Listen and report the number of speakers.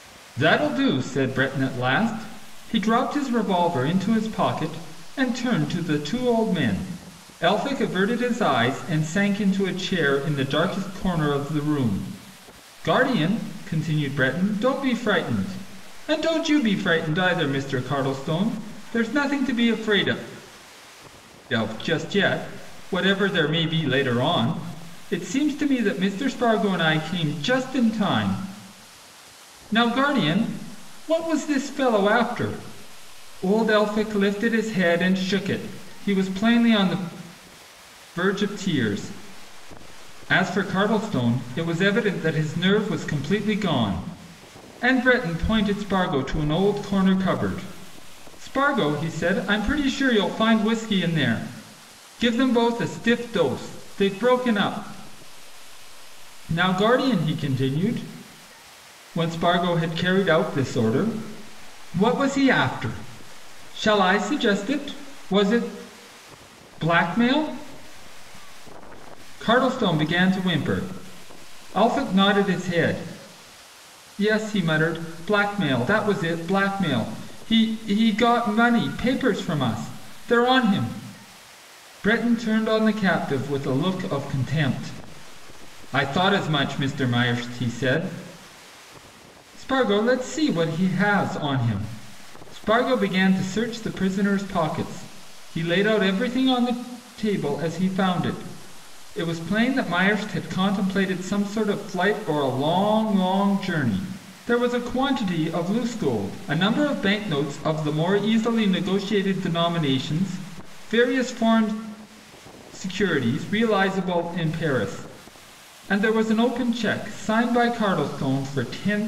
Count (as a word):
one